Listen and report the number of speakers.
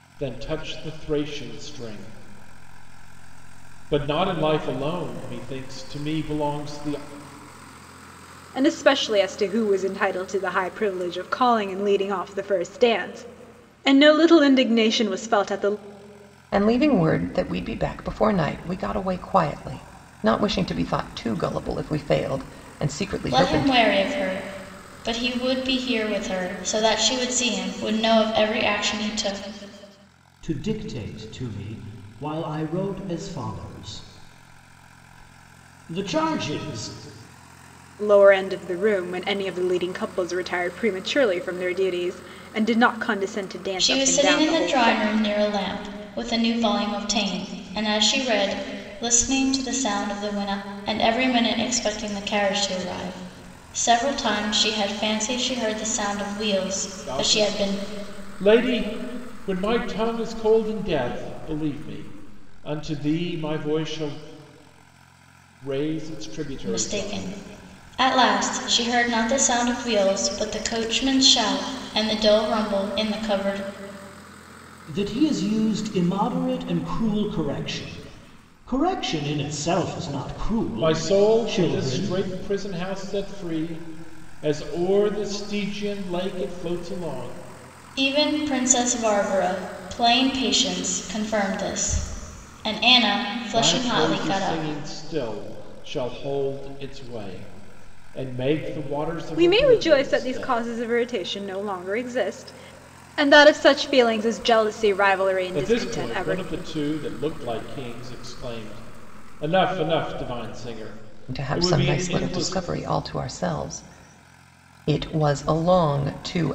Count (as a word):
five